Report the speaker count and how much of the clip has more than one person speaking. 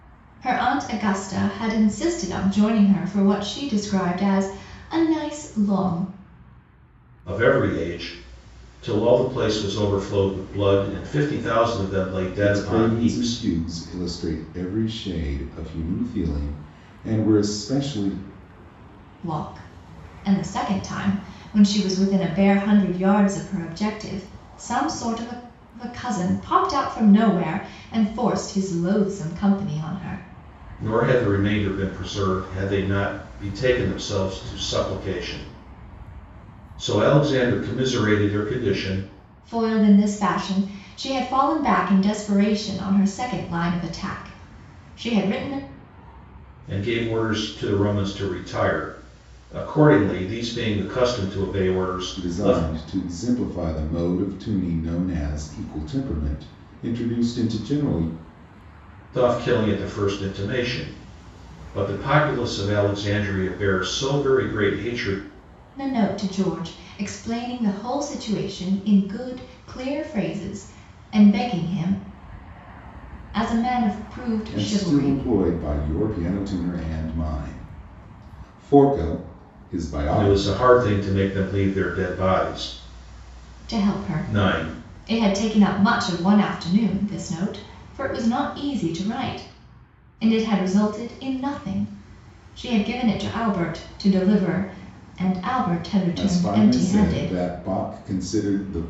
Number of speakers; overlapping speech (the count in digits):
3, about 5%